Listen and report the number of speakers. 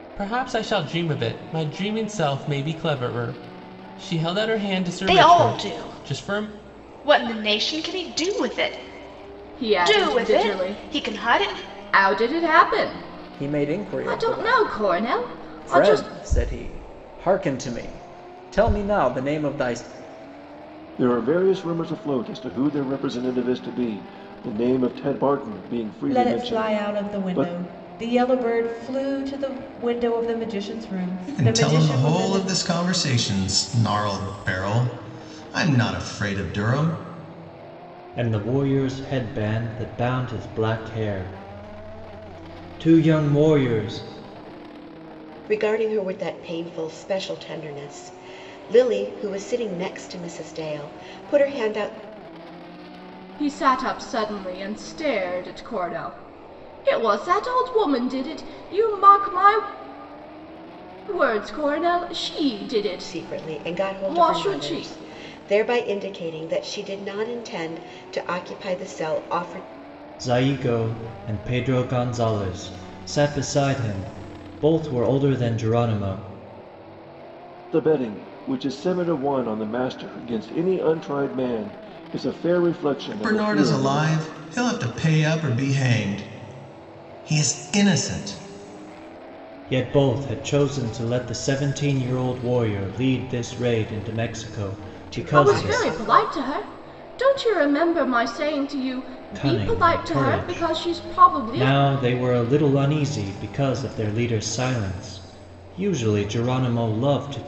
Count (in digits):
9